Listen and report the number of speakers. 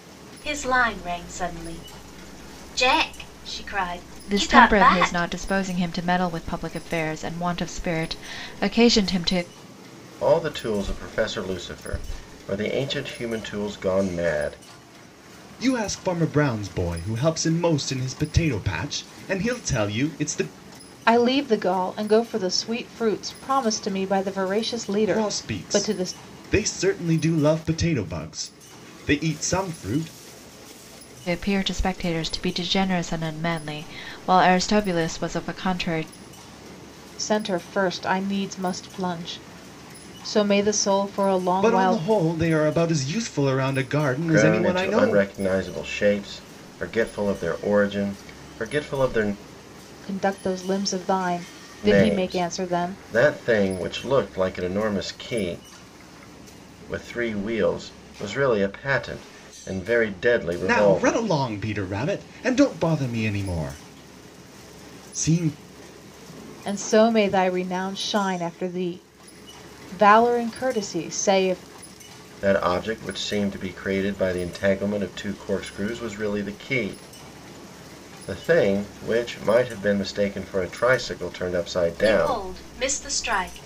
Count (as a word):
five